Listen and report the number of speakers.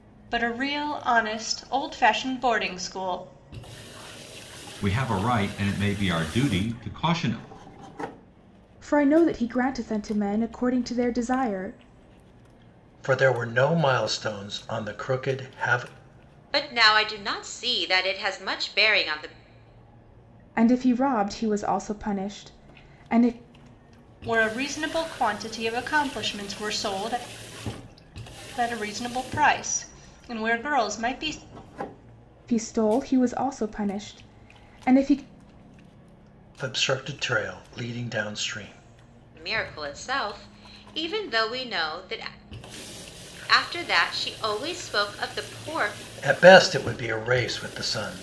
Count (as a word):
five